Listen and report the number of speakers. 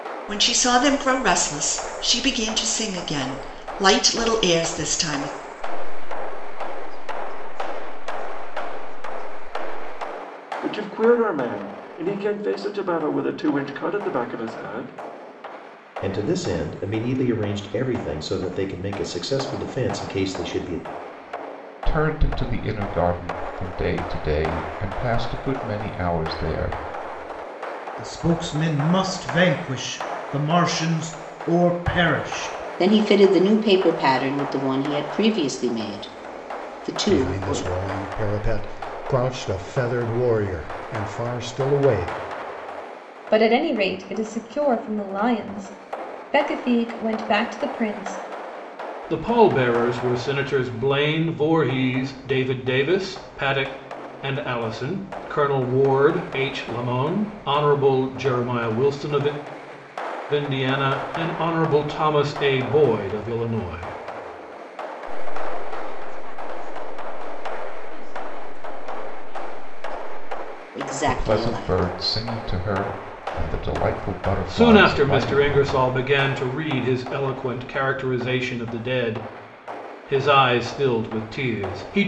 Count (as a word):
ten